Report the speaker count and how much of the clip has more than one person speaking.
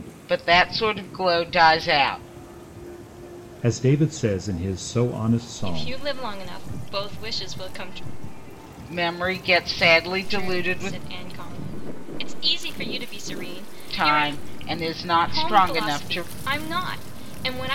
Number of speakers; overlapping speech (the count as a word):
three, about 15%